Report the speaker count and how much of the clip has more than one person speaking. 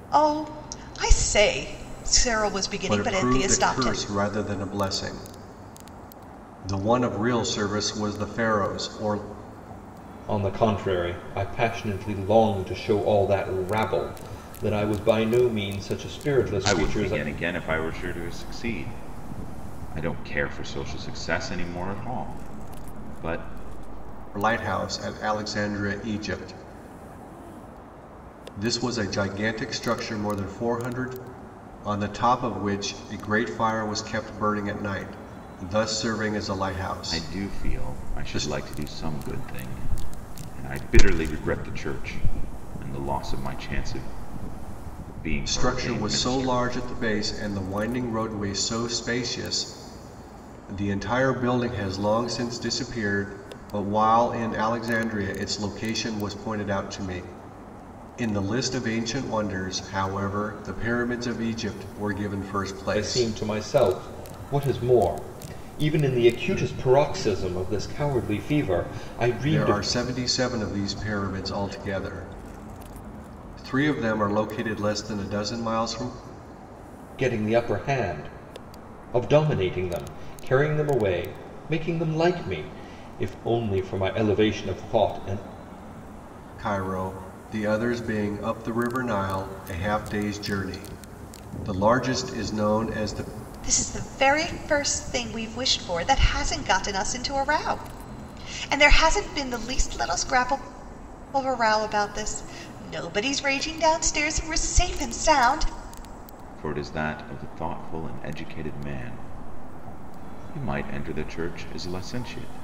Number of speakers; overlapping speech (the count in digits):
4, about 5%